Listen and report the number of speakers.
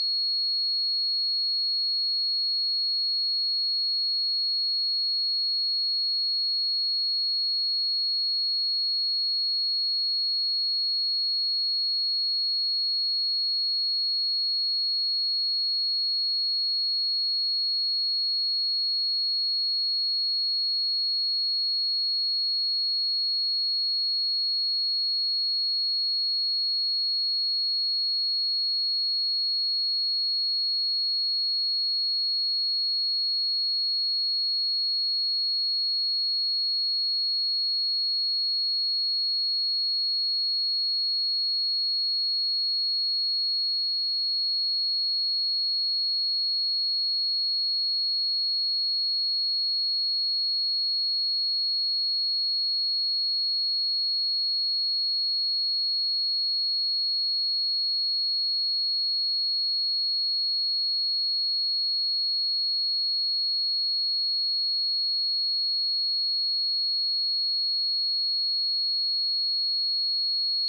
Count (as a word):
zero